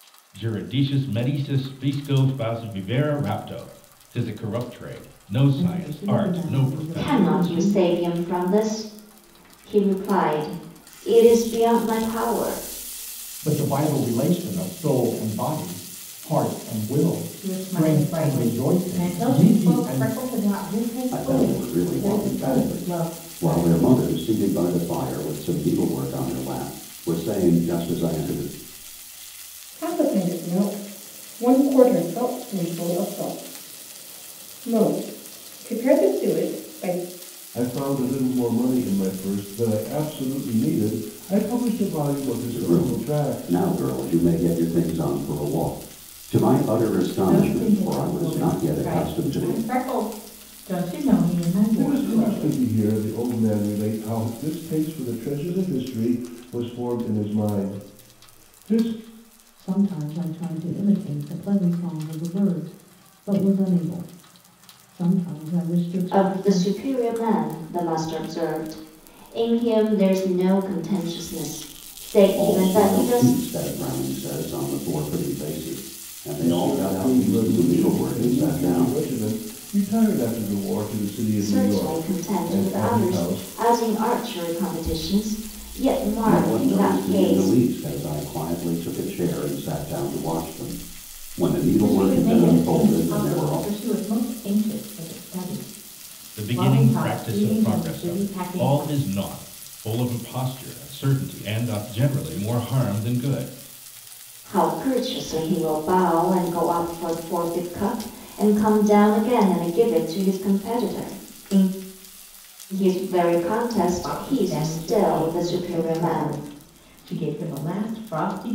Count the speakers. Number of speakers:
eight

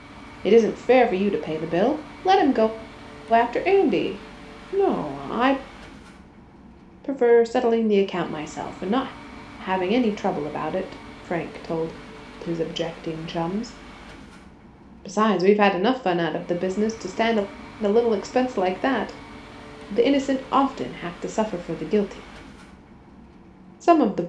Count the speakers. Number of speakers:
one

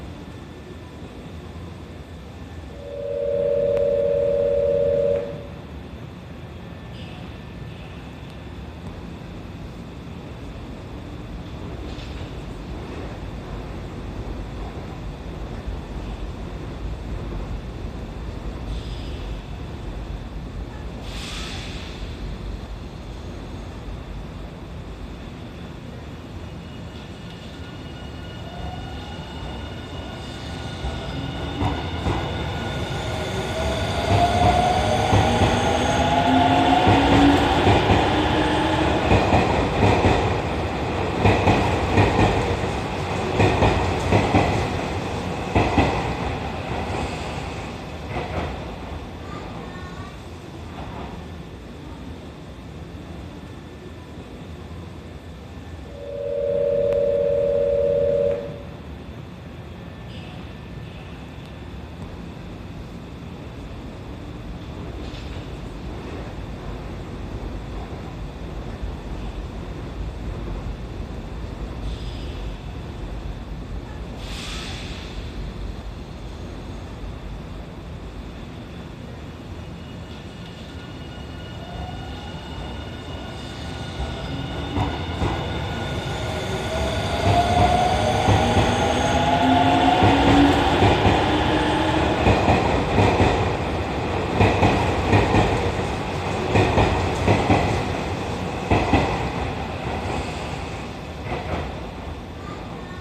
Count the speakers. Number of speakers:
zero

